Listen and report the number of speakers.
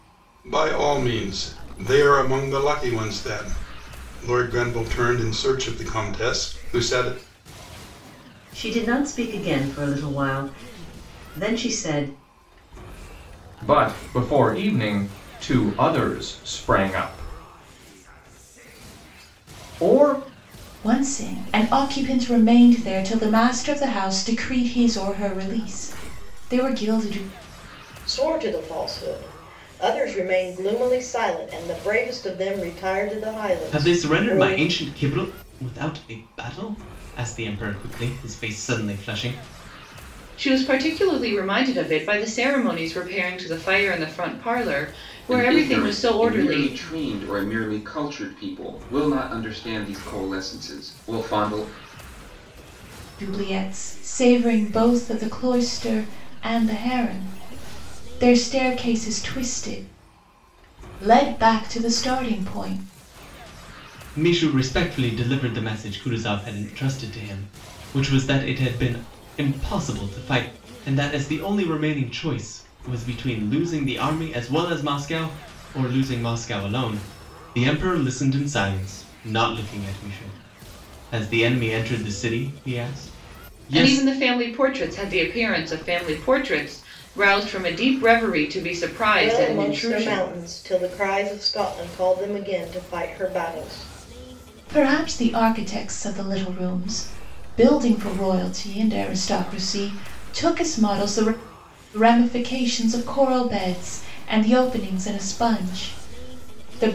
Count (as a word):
eight